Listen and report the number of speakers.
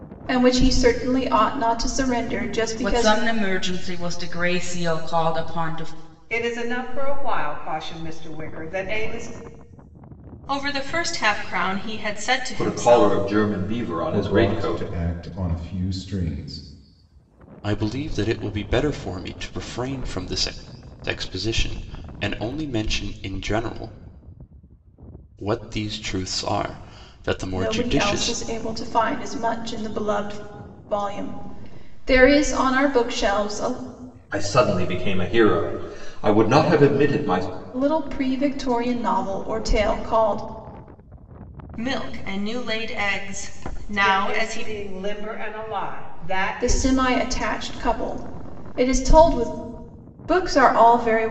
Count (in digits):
7